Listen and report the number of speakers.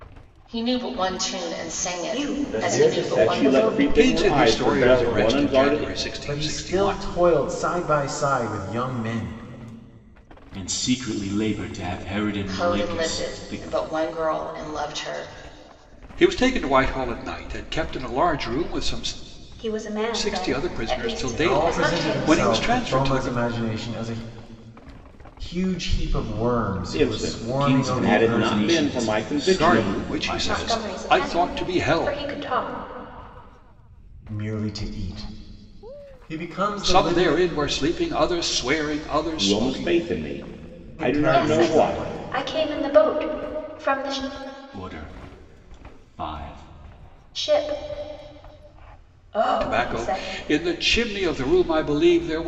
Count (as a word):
seven